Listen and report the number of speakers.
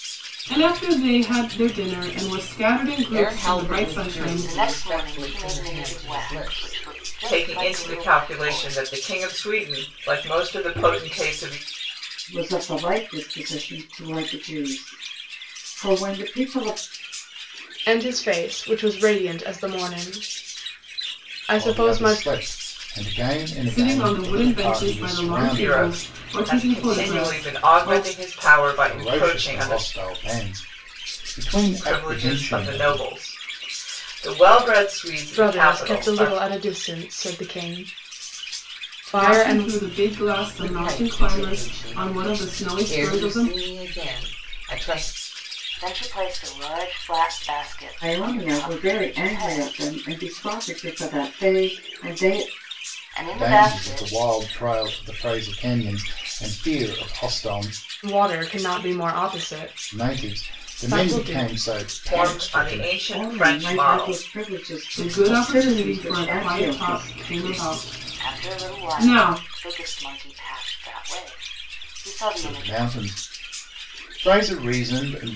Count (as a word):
seven